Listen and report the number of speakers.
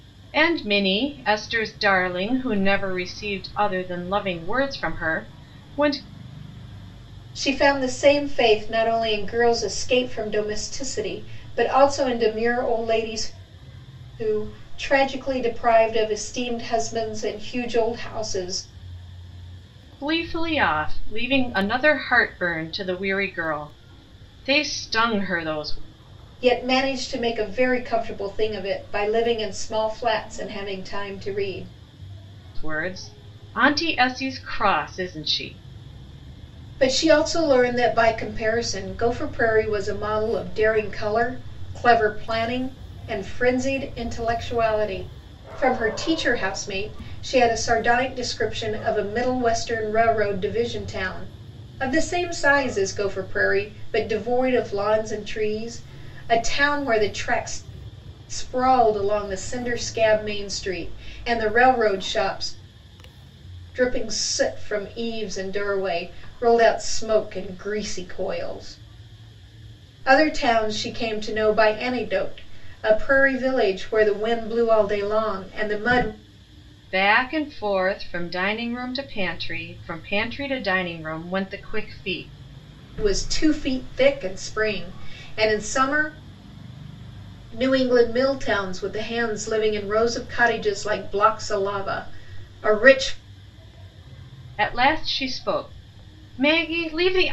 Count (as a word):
two